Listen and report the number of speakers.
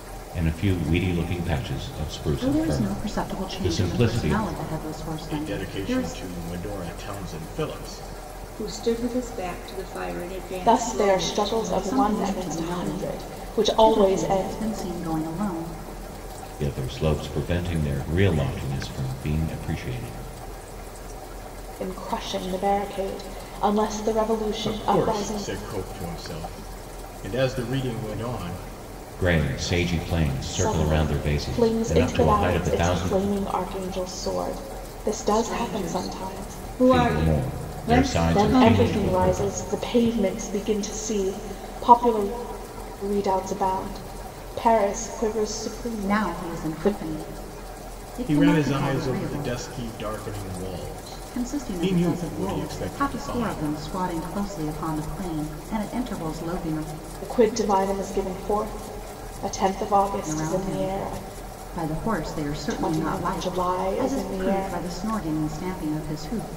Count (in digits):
5